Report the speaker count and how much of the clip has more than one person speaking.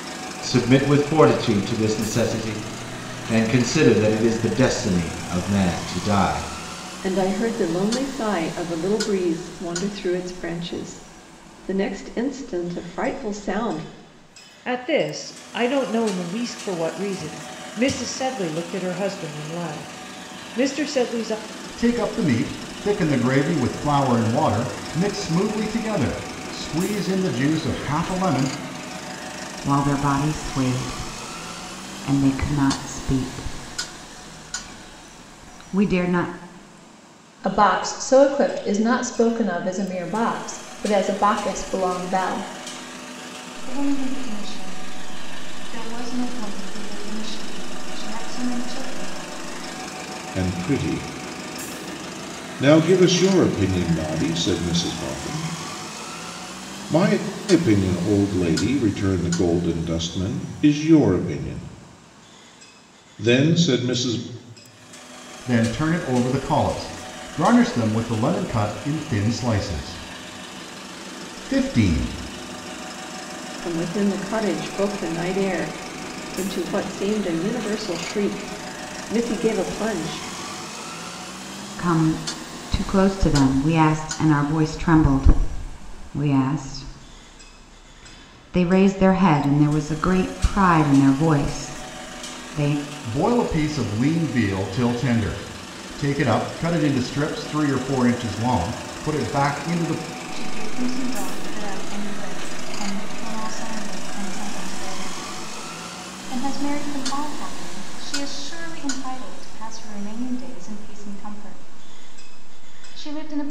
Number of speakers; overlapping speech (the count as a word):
eight, no overlap